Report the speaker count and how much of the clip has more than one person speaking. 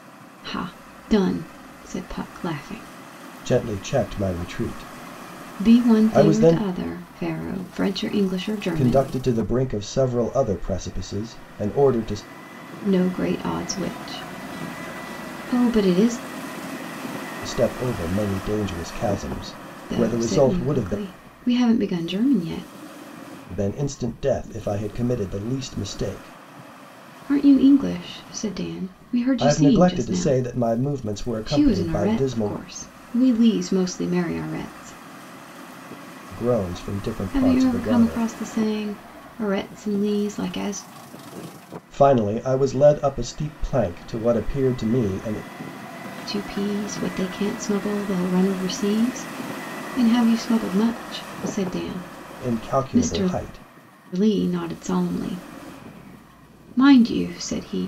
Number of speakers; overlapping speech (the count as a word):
two, about 12%